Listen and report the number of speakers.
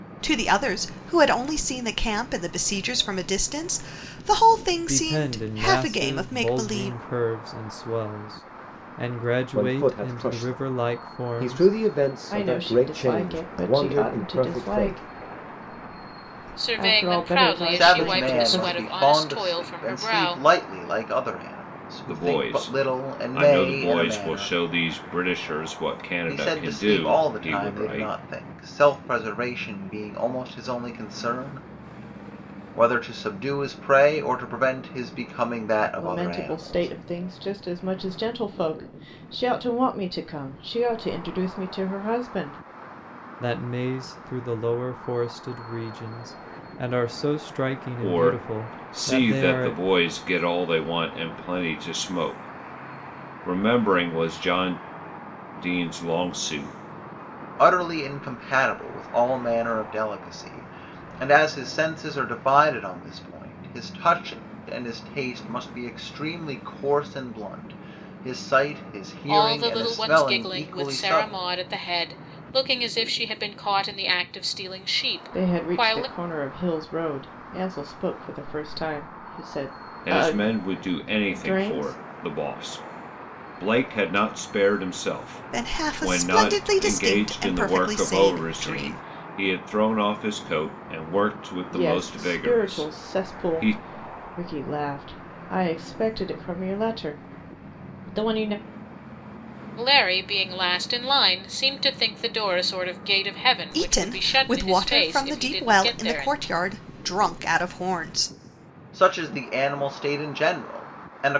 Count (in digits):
7